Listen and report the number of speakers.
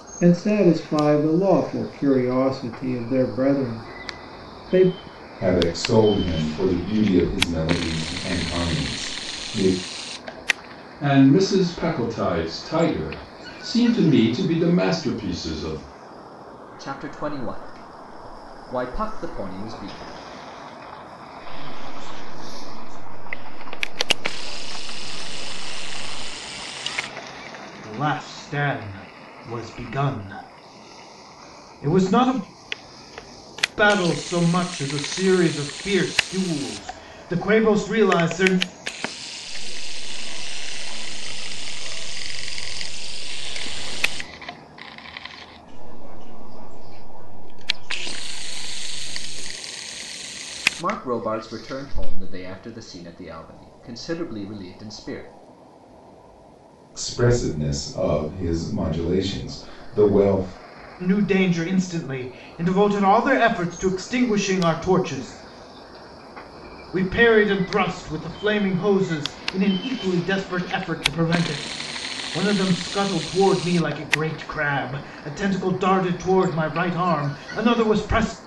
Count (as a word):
six